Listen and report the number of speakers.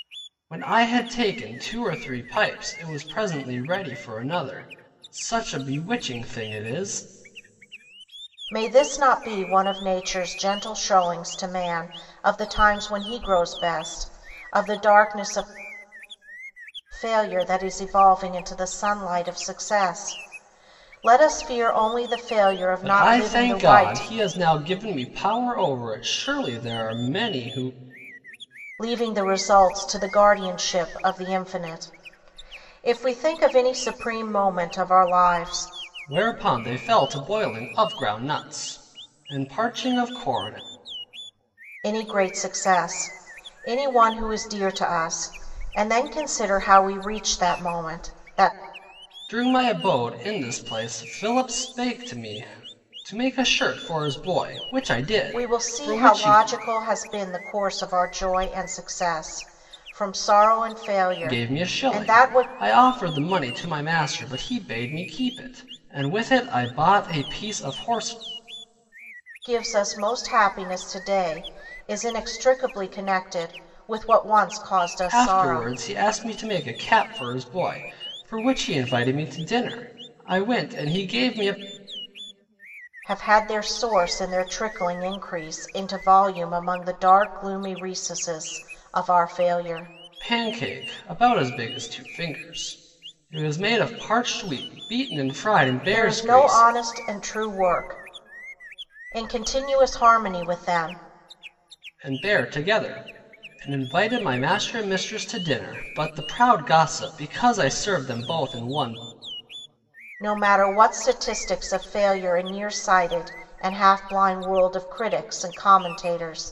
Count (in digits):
2